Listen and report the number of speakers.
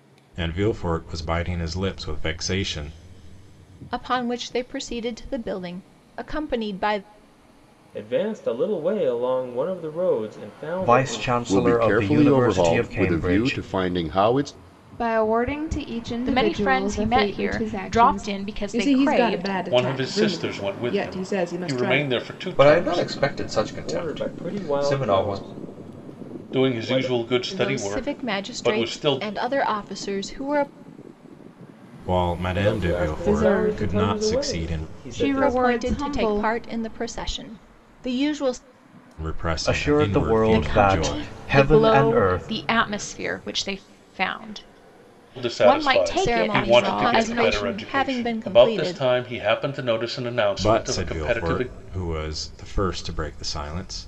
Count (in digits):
10